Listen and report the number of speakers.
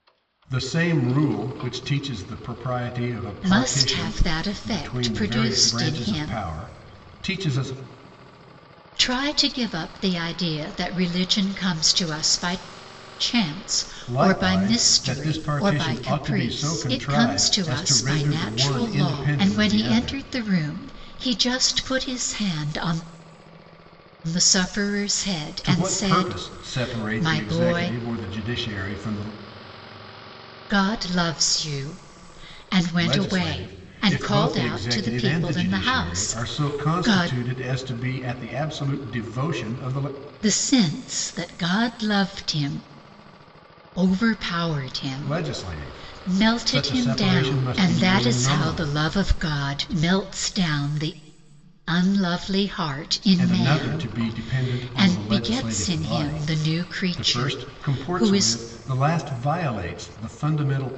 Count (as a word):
two